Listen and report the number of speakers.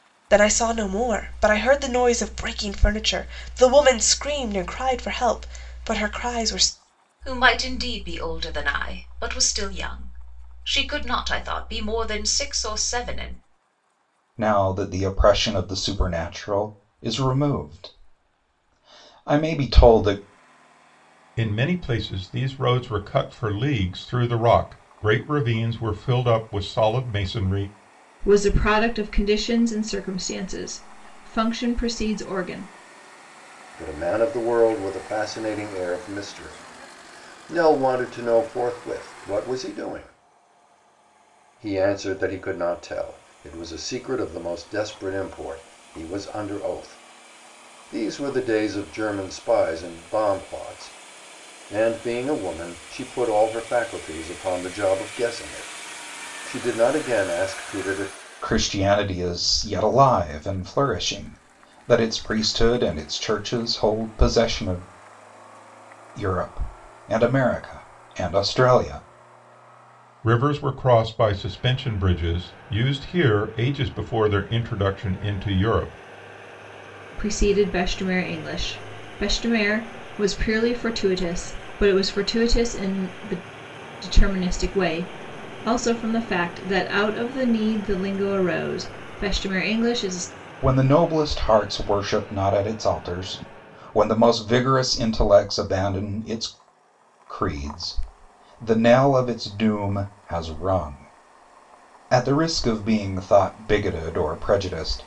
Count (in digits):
6